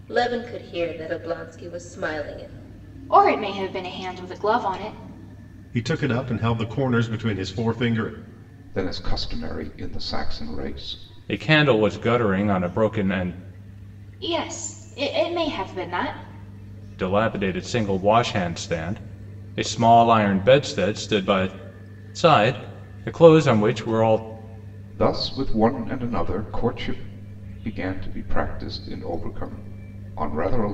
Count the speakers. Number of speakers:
five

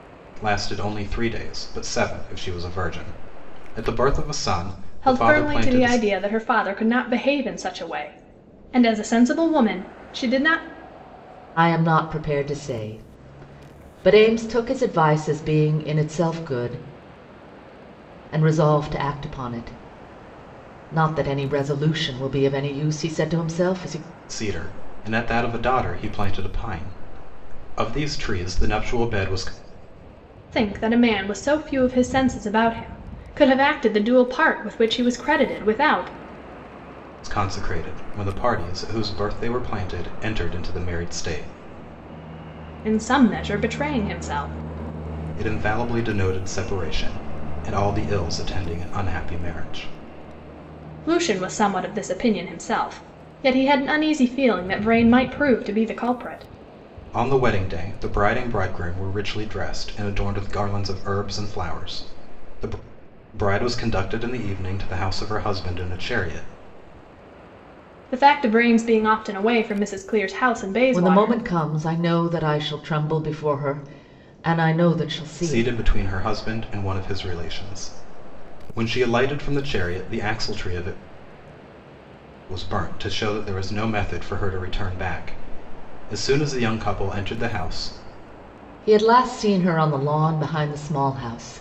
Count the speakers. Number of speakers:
three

